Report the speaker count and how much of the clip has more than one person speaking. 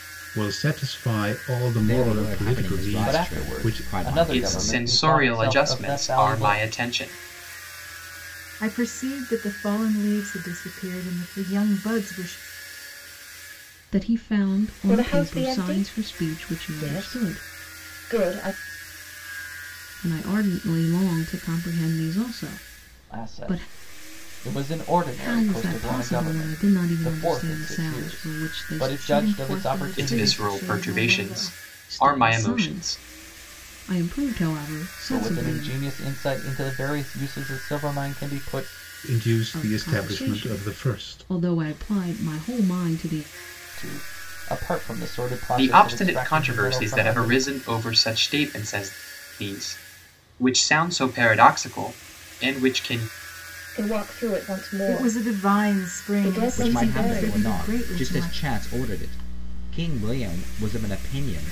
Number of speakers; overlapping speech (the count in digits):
7, about 38%